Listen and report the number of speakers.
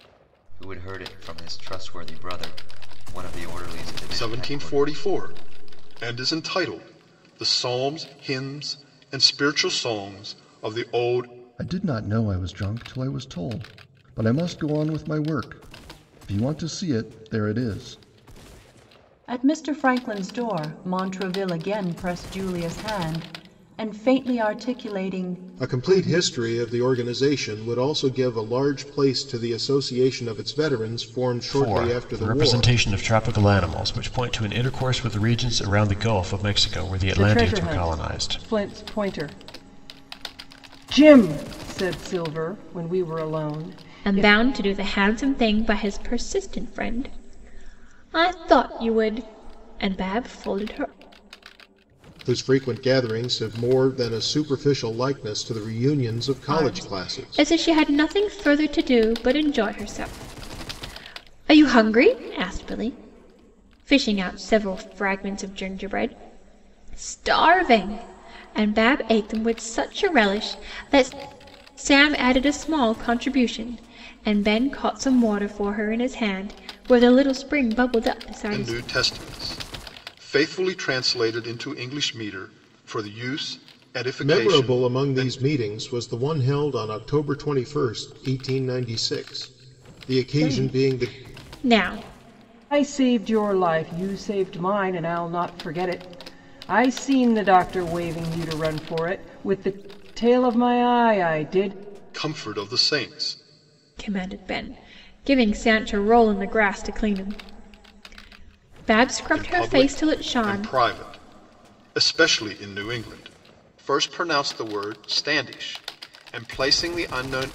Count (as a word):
eight